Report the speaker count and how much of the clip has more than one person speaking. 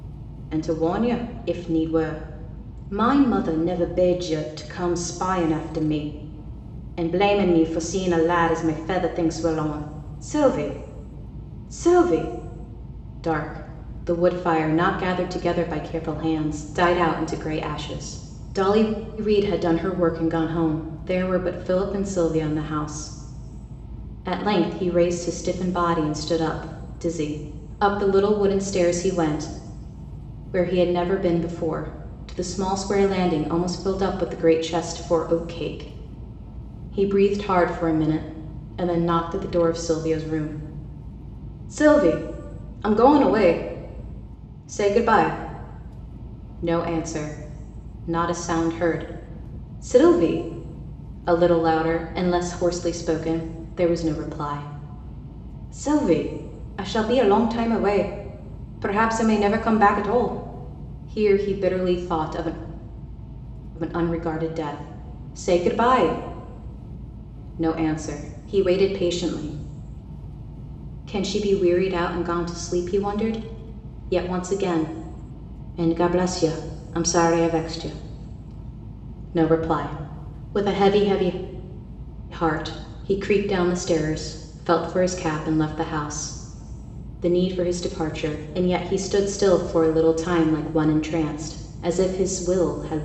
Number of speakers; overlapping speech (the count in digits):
1, no overlap